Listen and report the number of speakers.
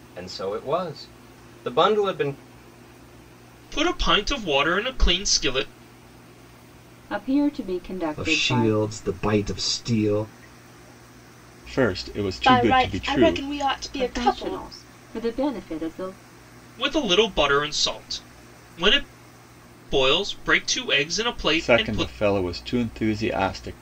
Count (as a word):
six